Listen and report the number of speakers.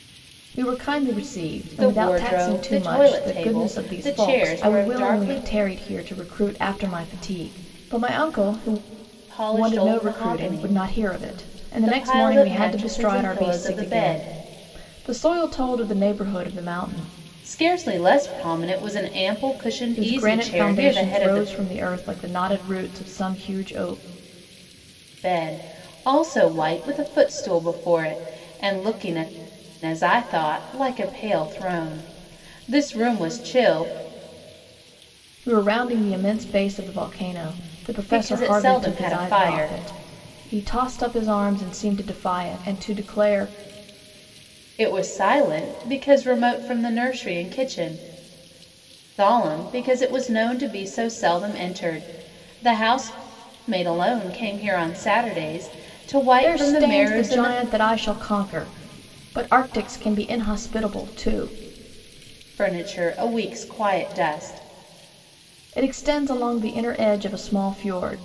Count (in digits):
2